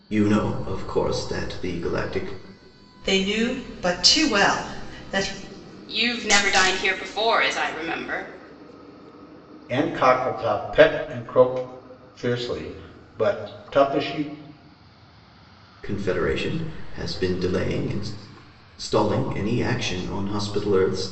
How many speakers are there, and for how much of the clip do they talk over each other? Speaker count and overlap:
four, no overlap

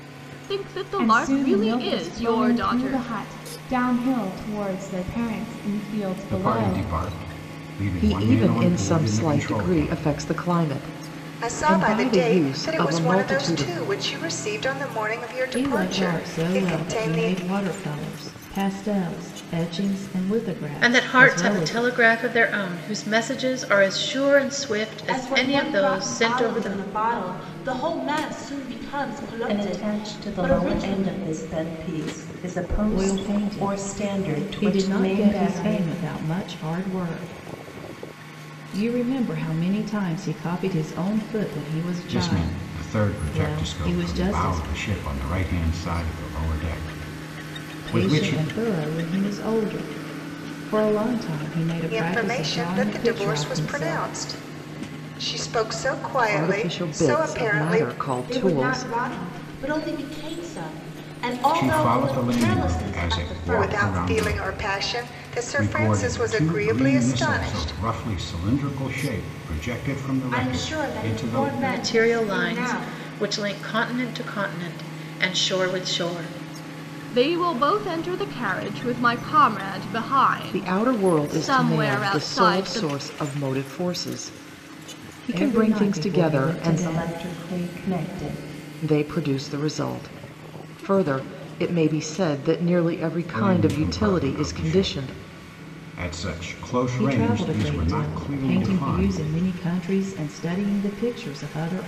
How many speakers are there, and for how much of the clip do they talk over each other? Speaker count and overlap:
nine, about 40%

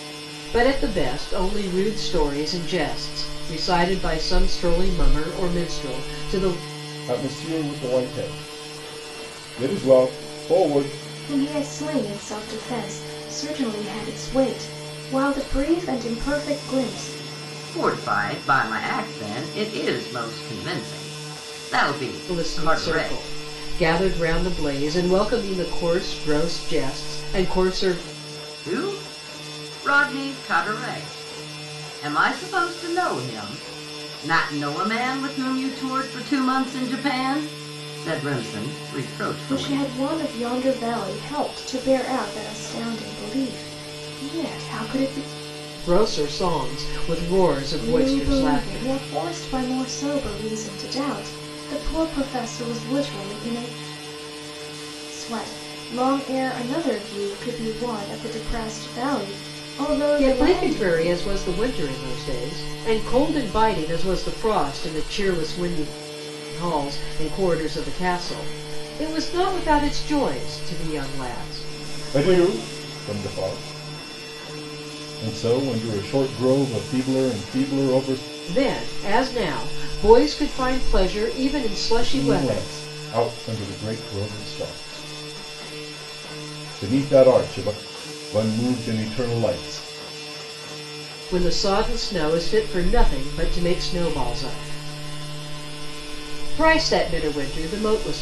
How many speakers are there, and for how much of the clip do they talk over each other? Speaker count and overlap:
four, about 5%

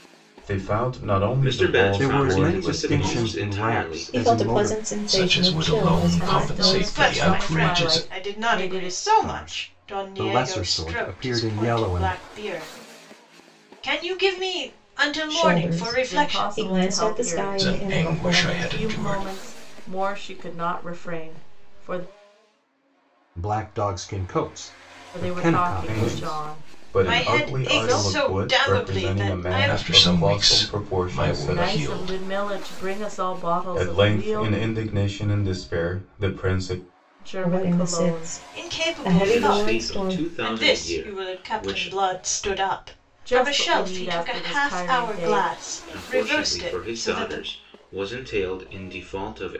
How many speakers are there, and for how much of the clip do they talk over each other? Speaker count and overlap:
seven, about 61%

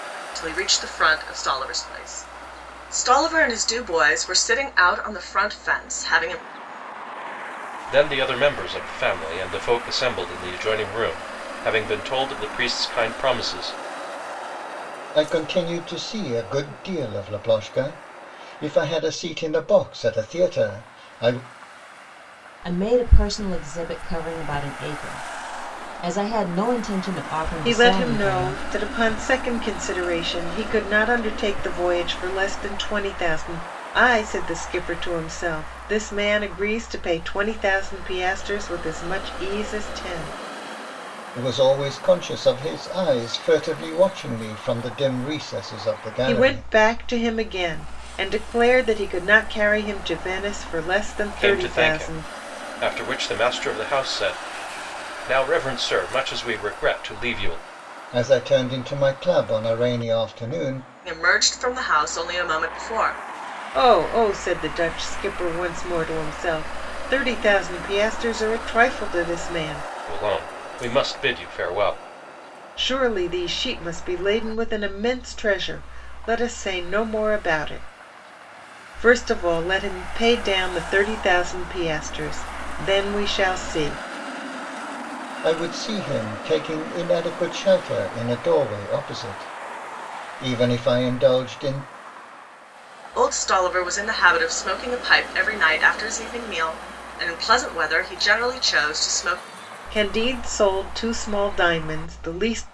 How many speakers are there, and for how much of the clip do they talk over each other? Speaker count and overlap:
five, about 2%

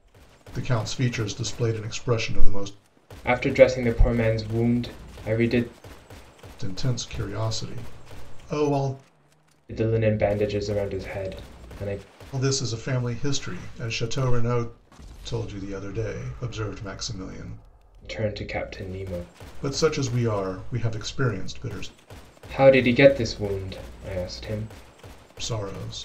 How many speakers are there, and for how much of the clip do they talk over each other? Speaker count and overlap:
two, no overlap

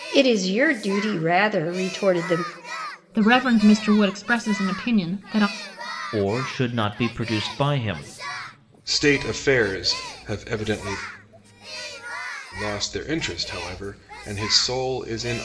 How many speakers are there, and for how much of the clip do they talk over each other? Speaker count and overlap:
four, no overlap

